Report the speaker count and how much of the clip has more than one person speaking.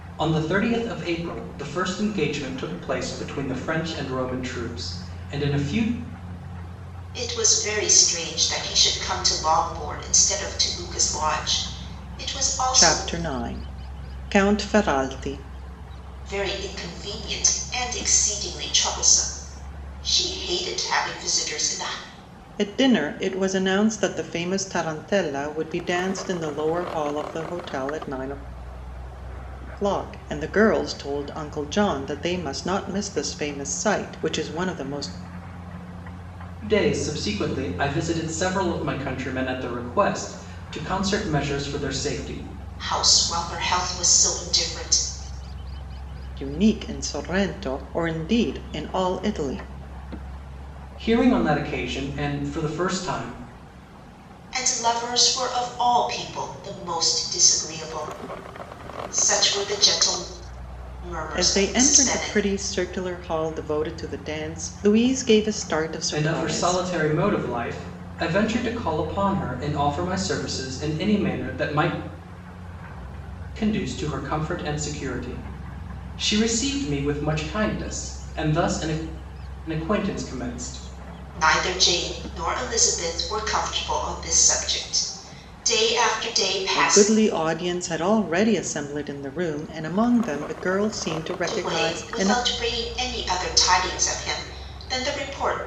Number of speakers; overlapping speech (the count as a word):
three, about 4%